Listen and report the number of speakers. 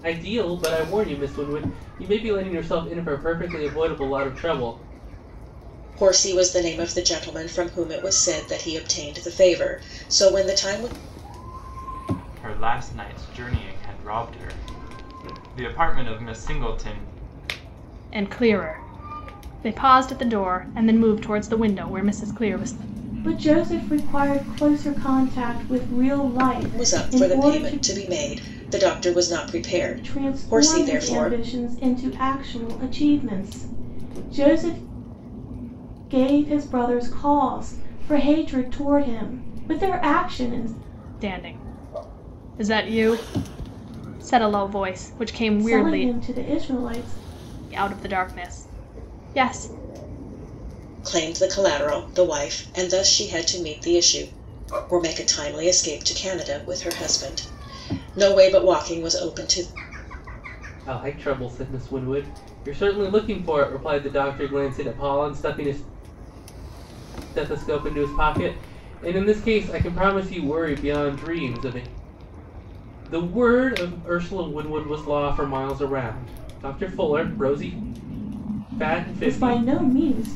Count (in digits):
5